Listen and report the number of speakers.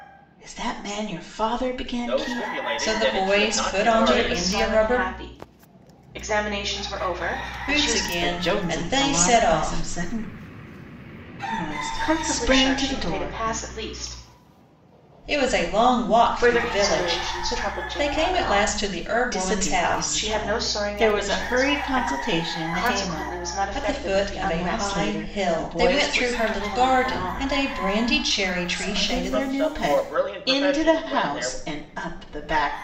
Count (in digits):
4